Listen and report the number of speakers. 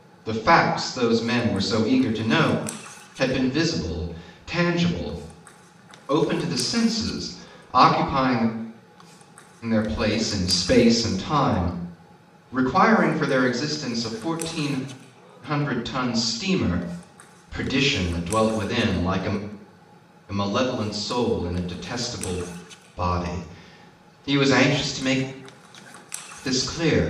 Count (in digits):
1